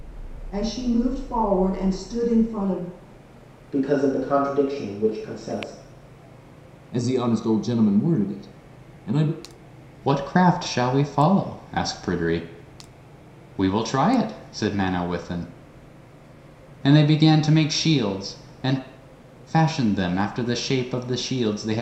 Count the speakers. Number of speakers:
4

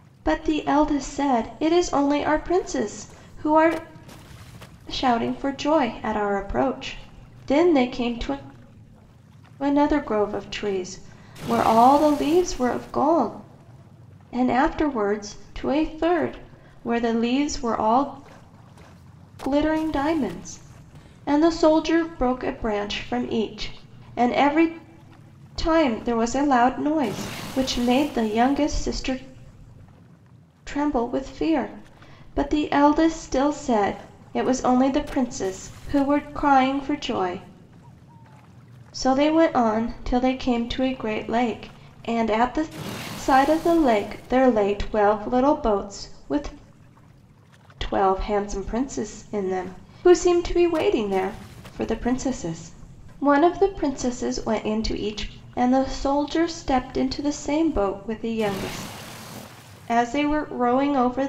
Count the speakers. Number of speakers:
1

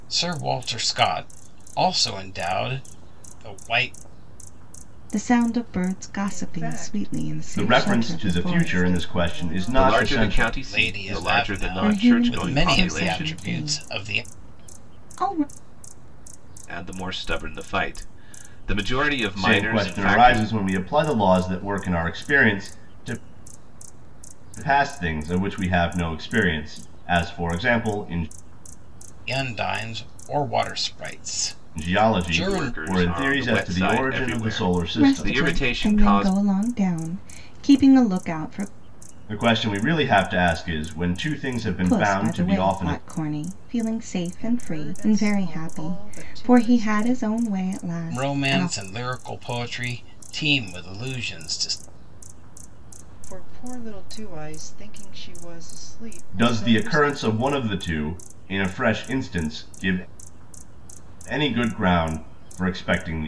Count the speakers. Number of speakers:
5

